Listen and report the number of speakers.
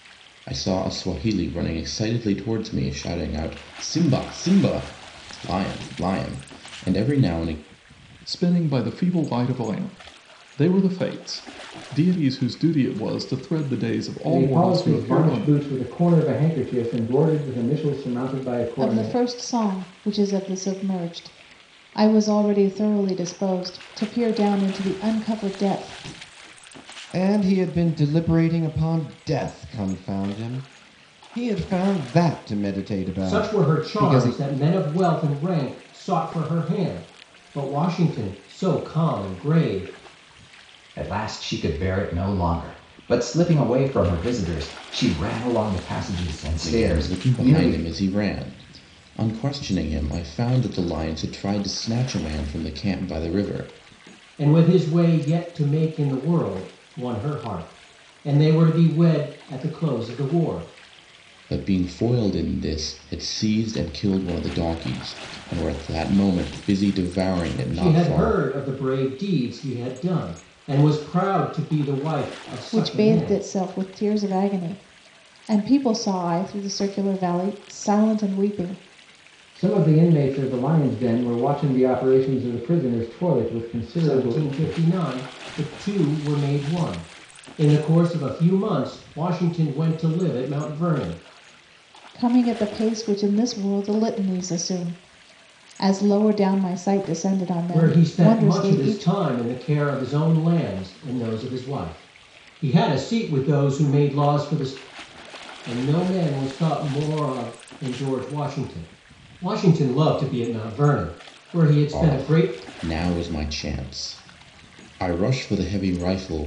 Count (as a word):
seven